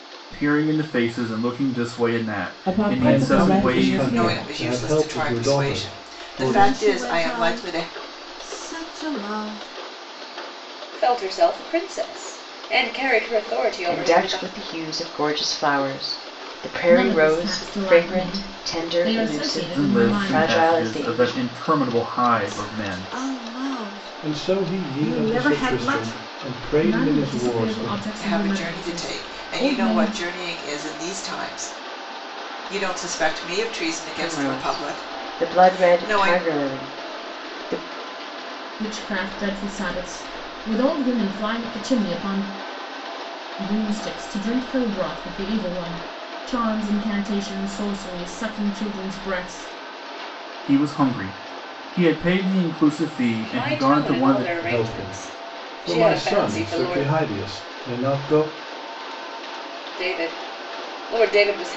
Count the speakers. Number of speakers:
8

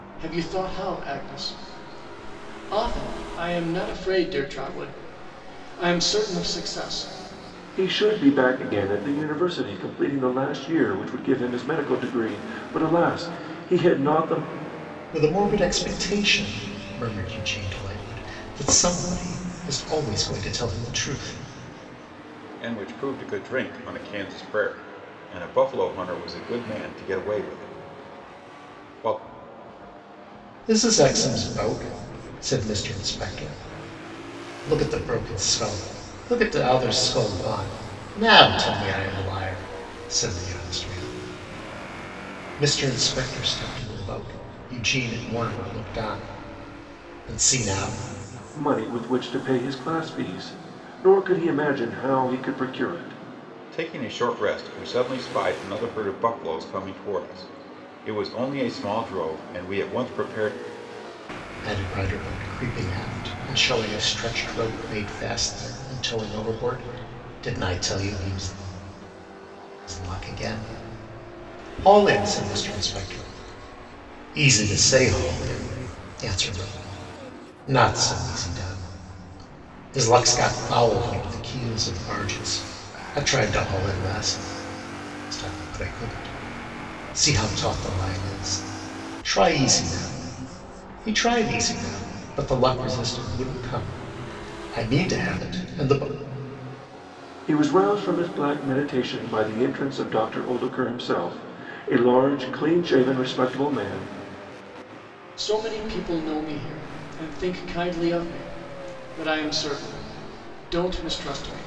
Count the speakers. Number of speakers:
4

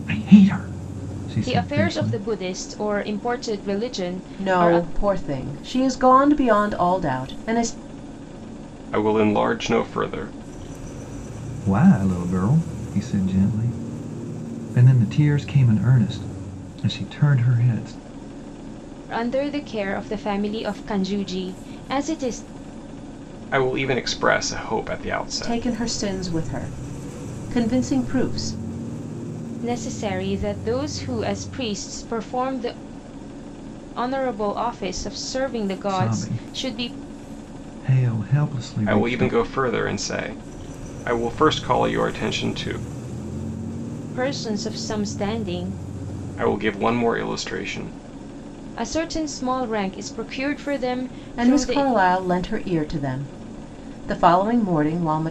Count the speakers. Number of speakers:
4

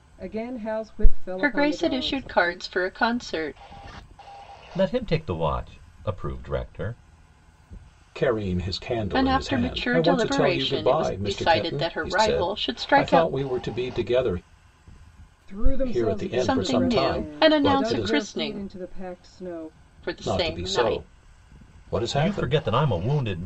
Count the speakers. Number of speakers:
4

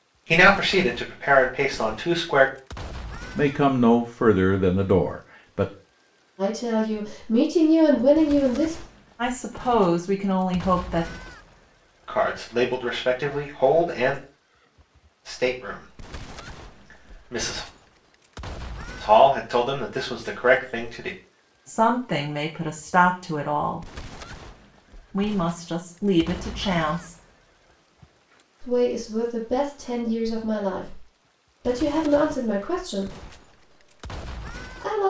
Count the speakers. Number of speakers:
4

